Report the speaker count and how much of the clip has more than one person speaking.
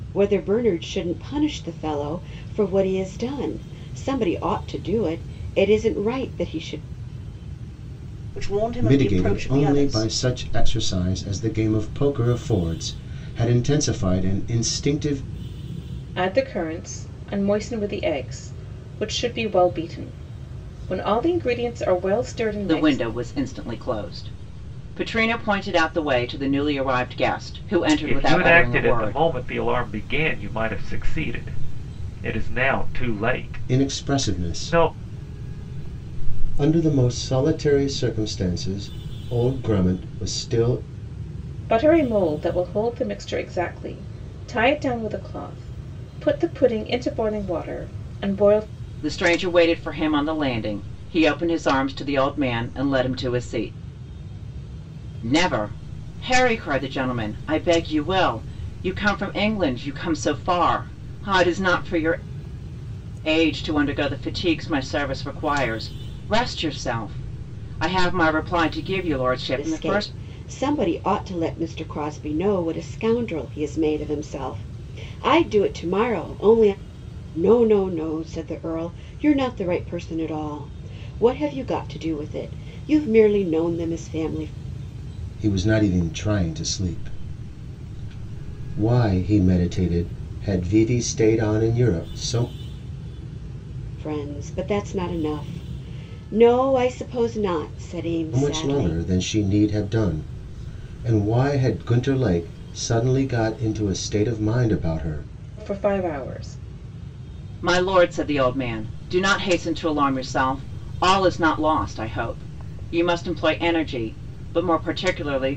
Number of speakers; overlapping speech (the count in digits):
6, about 5%